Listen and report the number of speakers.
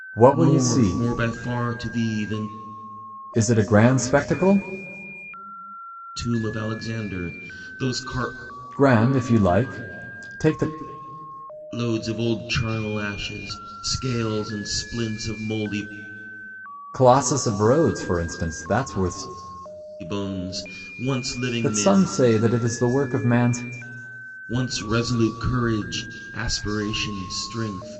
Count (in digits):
2